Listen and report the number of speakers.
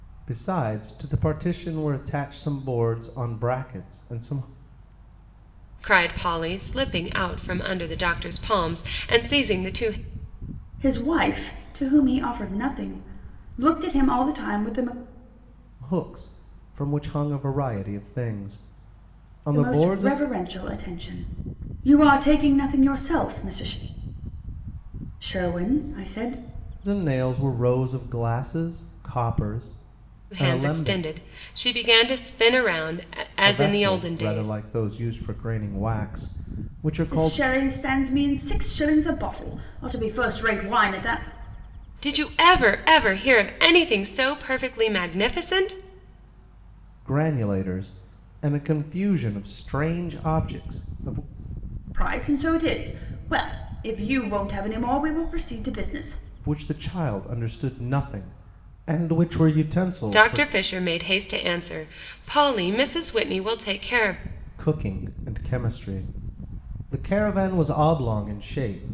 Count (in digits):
3